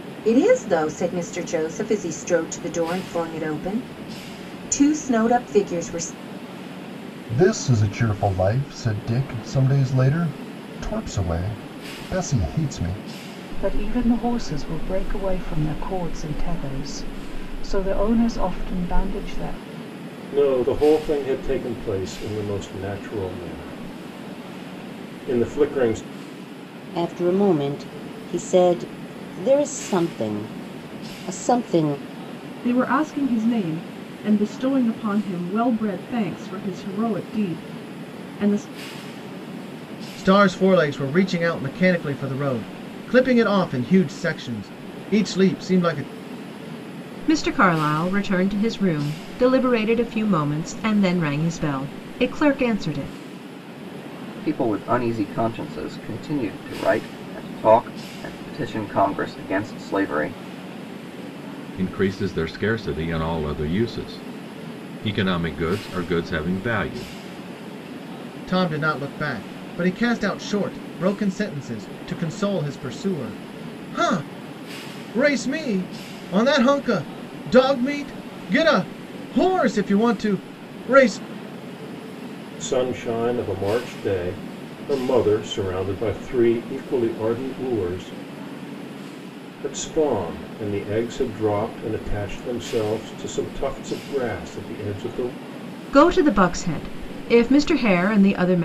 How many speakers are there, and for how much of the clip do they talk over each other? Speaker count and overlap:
10, no overlap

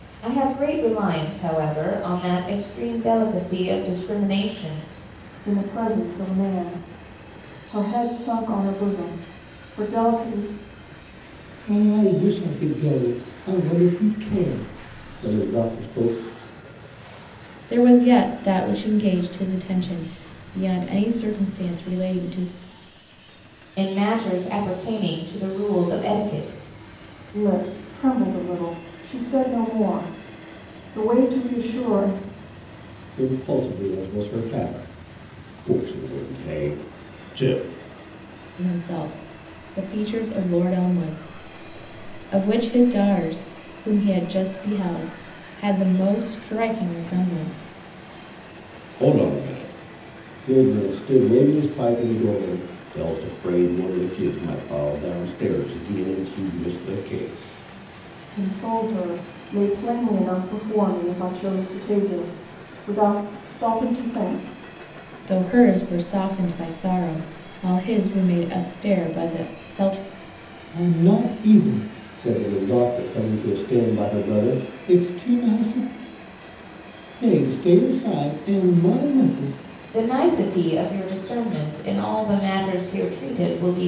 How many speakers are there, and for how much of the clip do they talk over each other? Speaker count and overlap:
4, no overlap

